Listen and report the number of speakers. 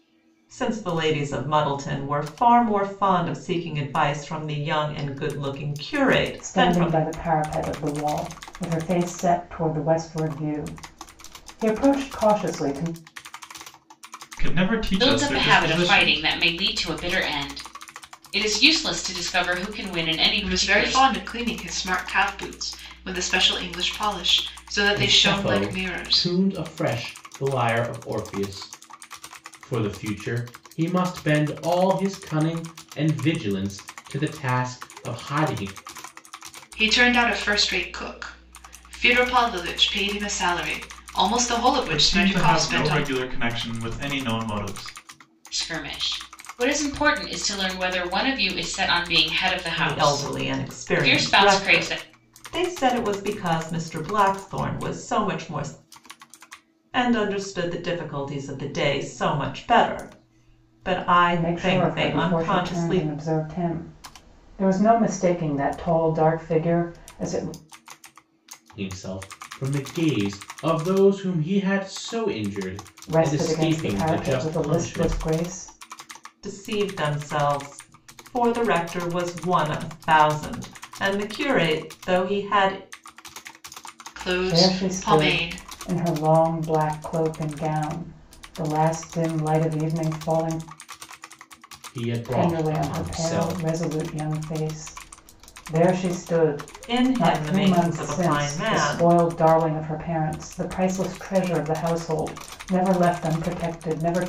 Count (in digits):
6